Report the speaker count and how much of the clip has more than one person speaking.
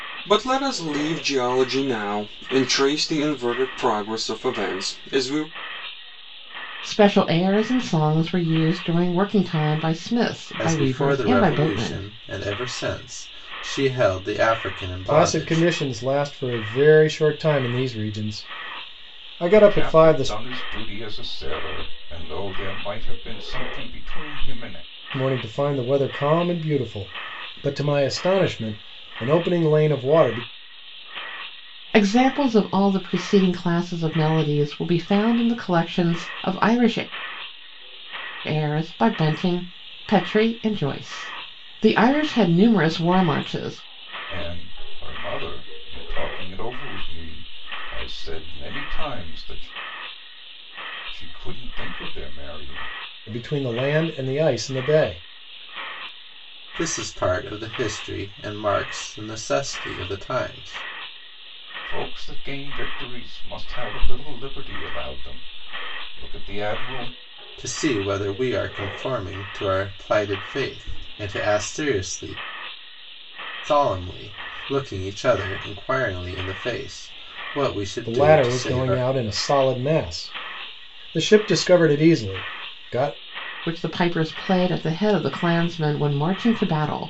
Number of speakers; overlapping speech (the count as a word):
five, about 5%